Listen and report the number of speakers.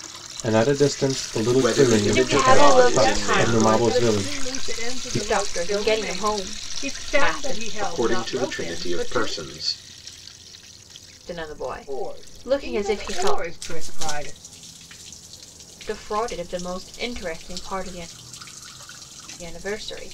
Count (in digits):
4